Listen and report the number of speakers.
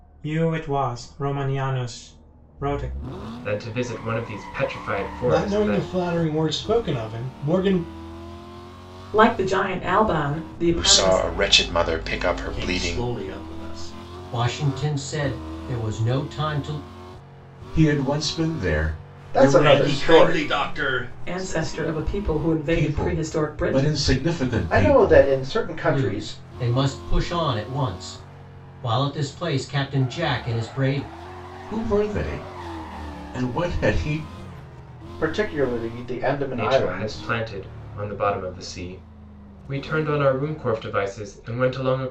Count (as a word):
nine